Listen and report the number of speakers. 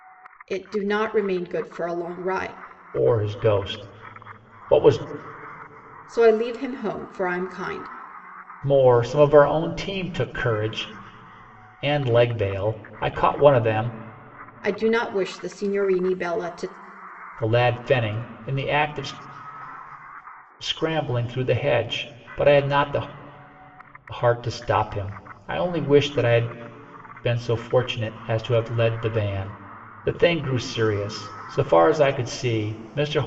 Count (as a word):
two